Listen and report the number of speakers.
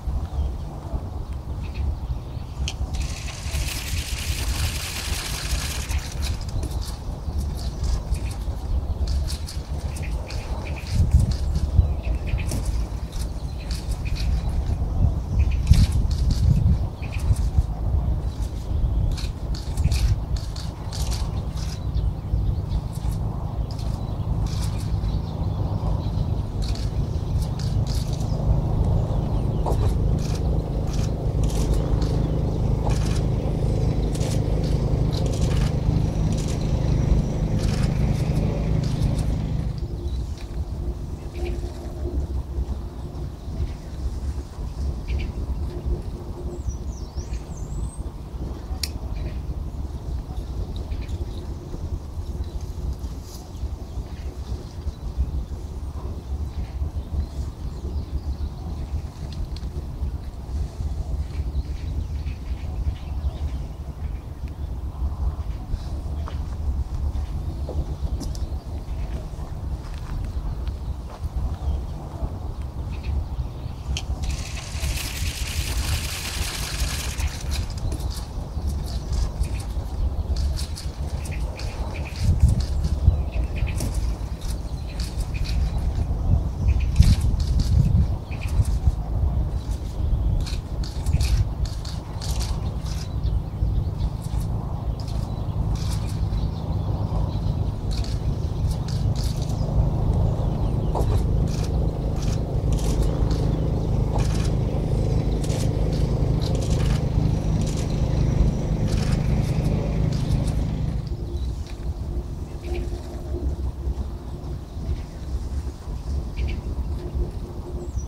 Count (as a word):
zero